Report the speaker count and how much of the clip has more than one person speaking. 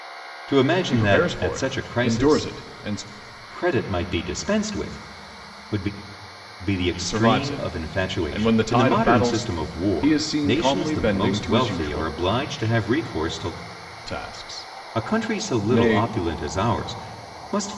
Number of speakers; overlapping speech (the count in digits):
2, about 42%